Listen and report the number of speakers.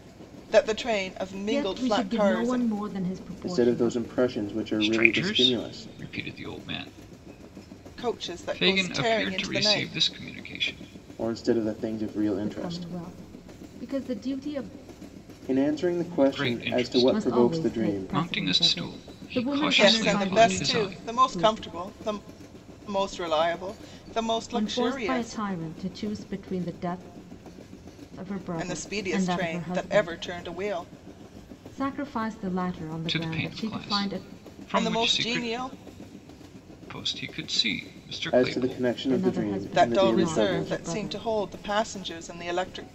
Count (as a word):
four